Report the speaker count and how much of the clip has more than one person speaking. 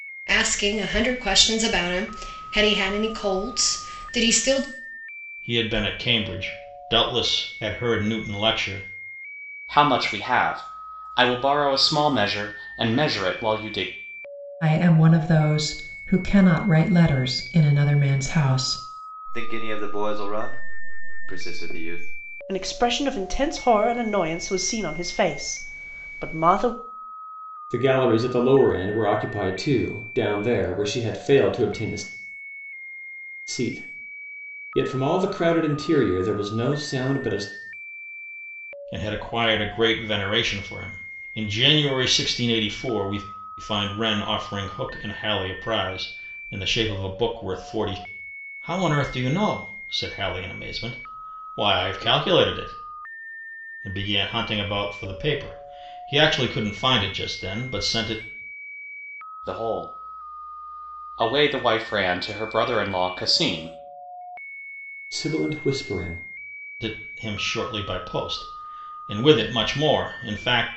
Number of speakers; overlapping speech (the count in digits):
7, no overlap